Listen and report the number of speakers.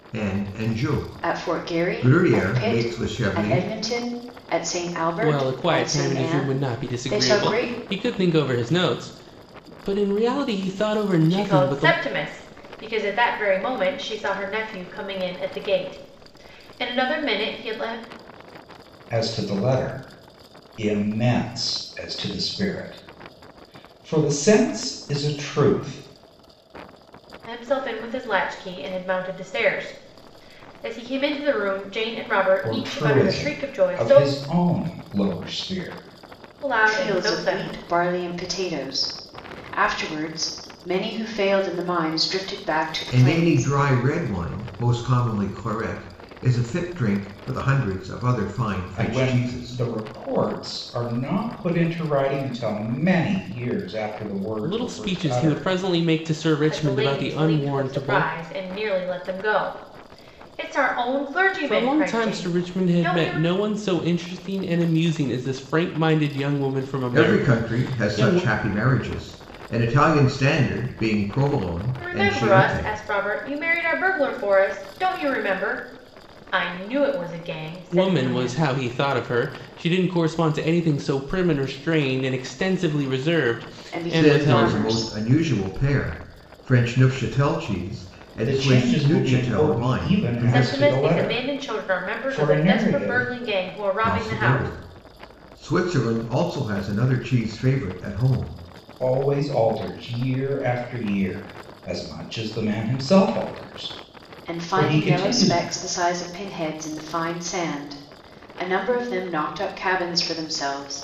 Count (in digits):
5